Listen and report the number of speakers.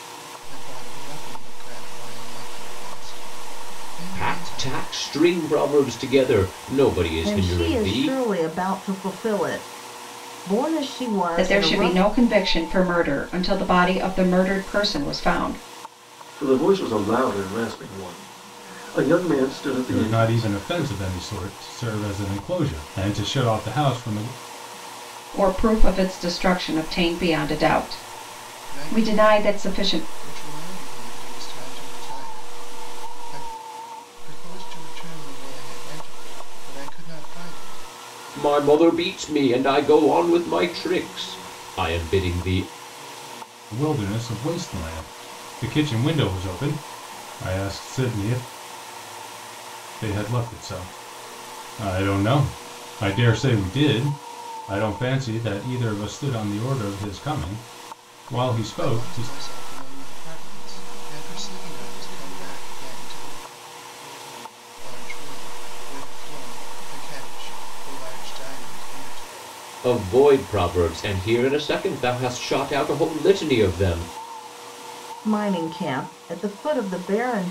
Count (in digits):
6